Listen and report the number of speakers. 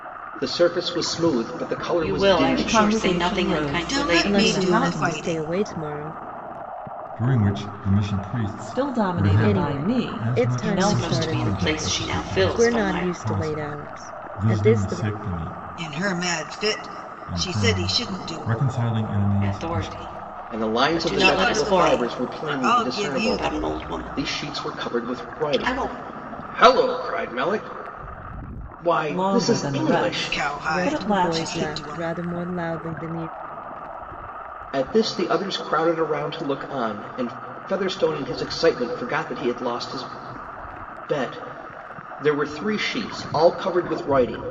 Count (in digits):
6